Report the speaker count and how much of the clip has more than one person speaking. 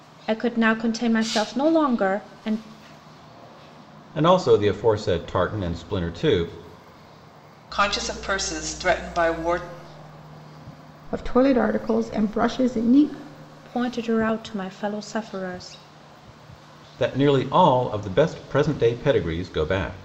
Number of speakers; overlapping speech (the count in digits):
4, no overlap